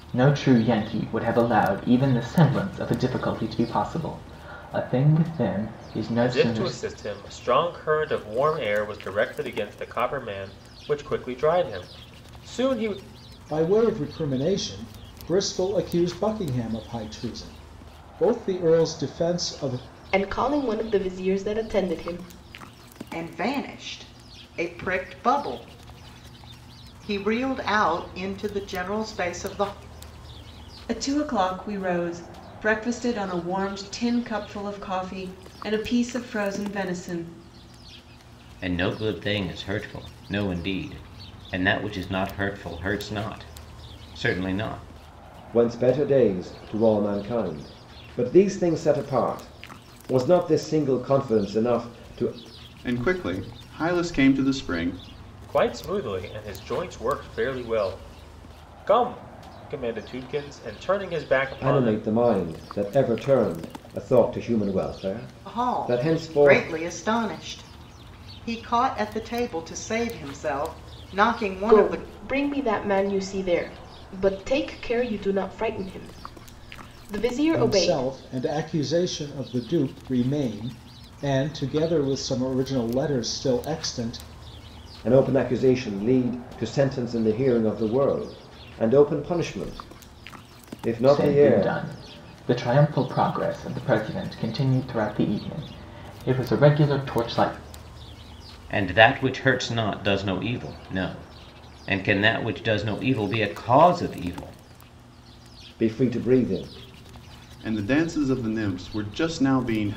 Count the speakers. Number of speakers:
9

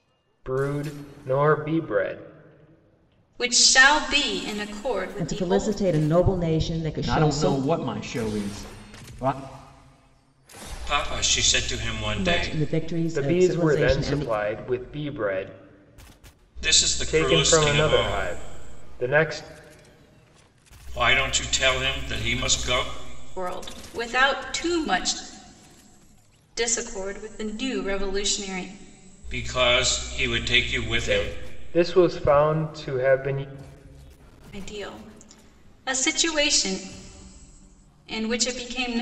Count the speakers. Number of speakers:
5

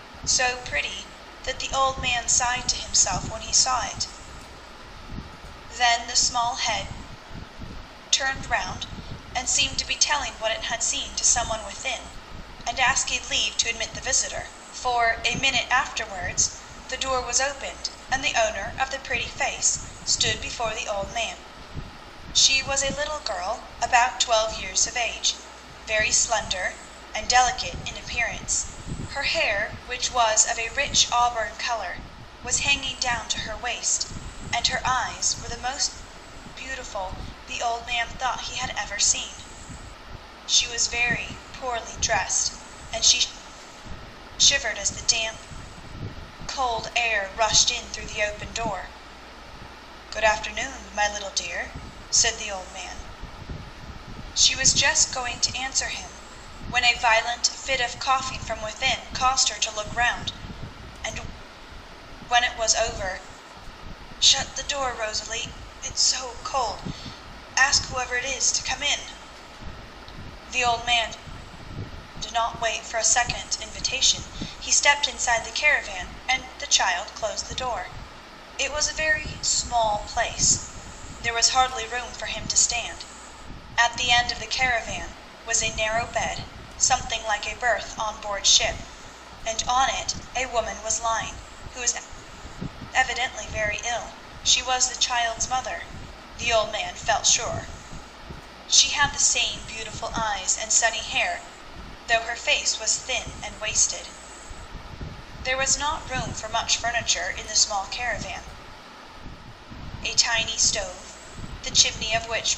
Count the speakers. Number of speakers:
1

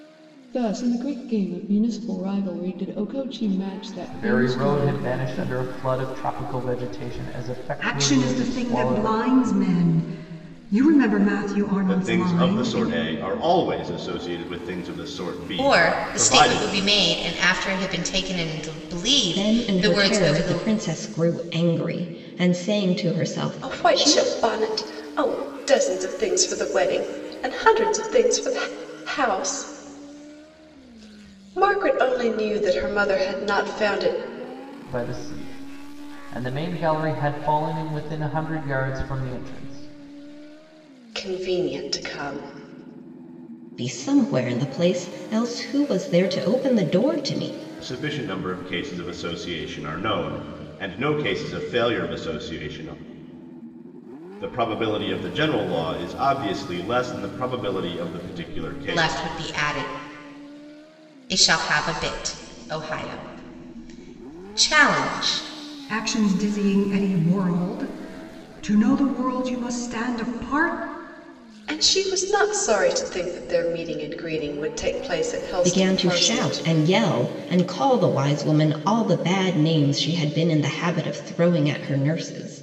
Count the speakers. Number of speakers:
7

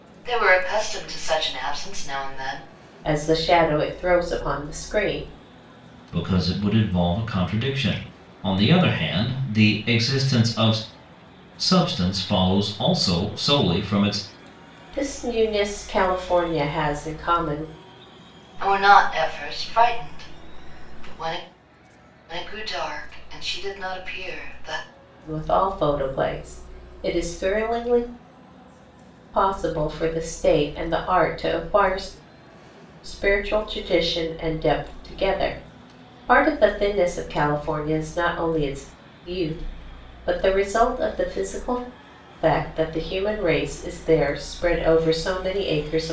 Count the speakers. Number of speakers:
3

